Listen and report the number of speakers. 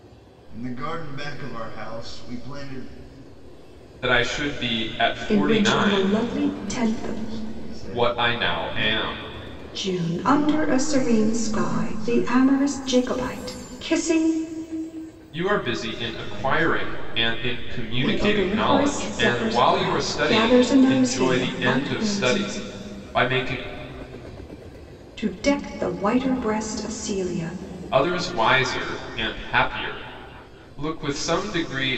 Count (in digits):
3